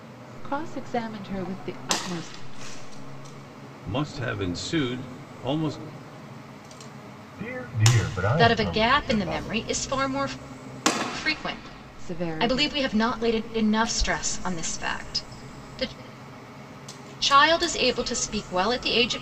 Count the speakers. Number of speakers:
4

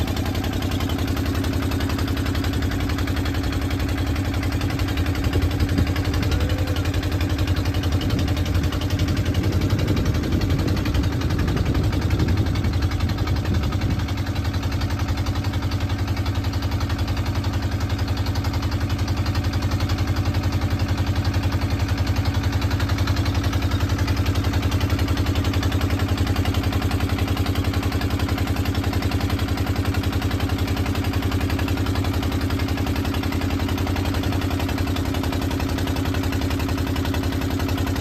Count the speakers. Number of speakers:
0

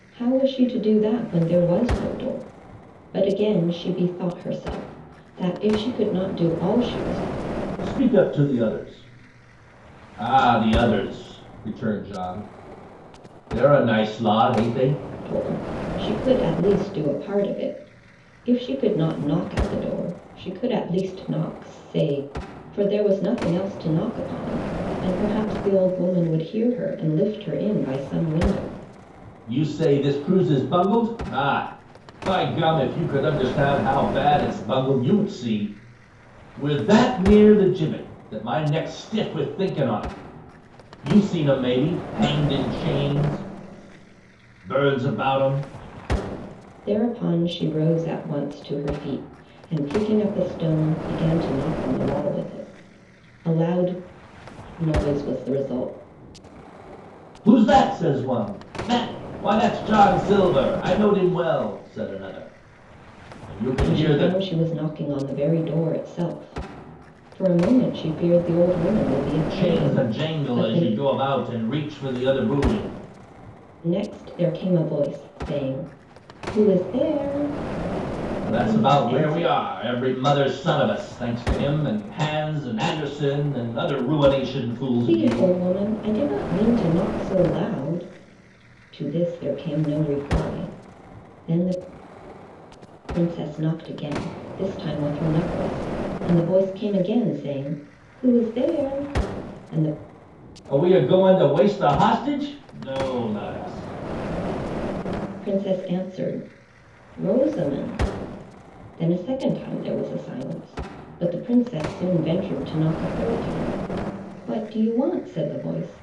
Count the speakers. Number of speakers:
2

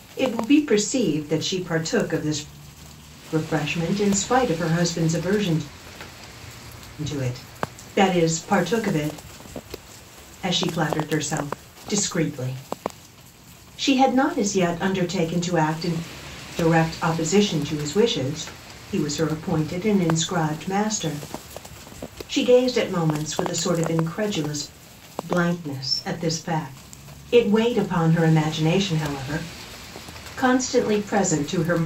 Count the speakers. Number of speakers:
1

